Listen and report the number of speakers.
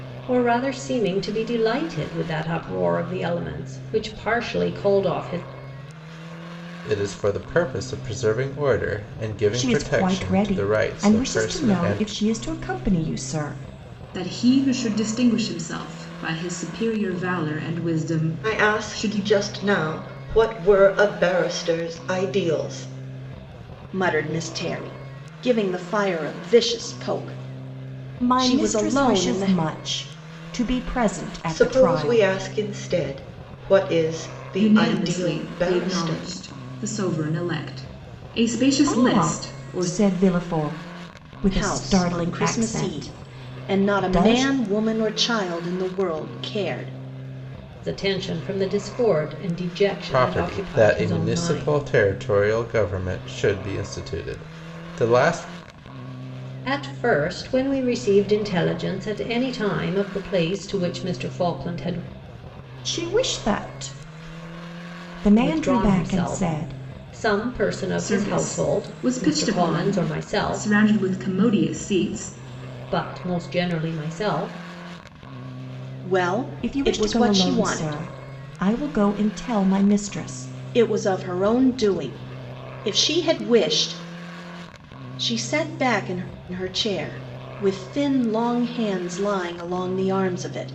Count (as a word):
six